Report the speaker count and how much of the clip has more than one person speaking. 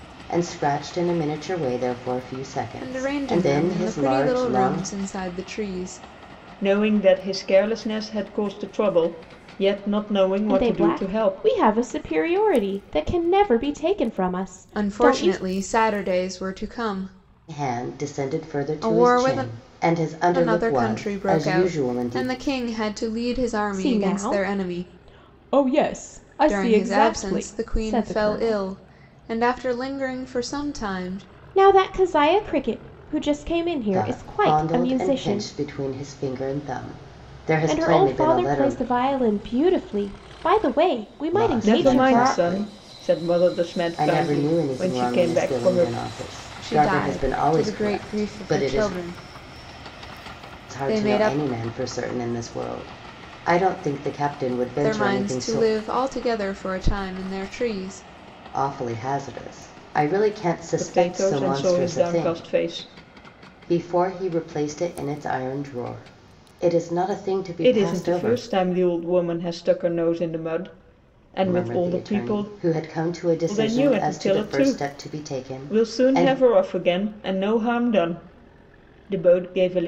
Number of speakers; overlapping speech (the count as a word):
four, about 35%